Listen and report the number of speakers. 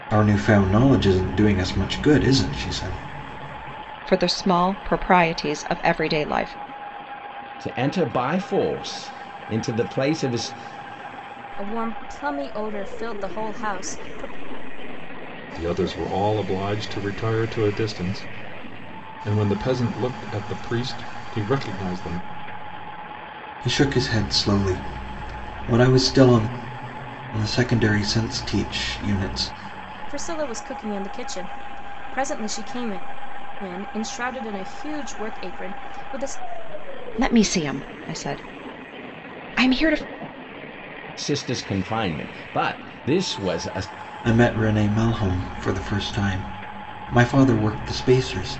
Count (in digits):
5